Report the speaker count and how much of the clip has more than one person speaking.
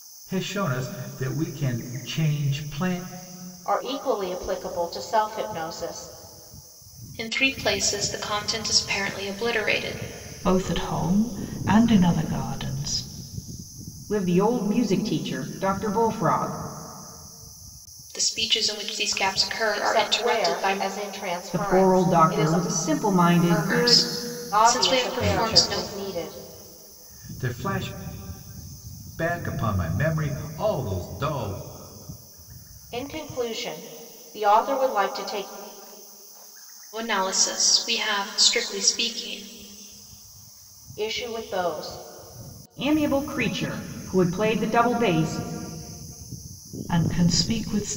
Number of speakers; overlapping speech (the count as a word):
five, about 10%